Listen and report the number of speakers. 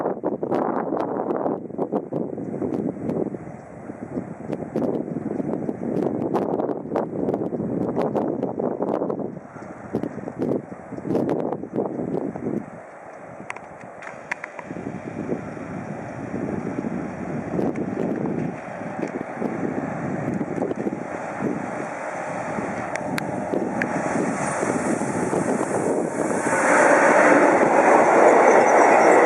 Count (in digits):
0